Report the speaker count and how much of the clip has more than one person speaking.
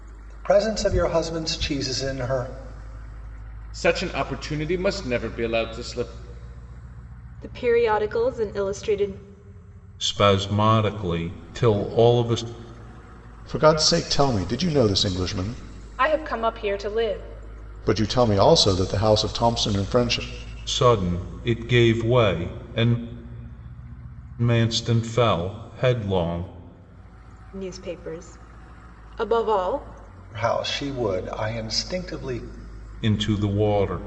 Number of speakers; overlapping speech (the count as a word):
six, no overlap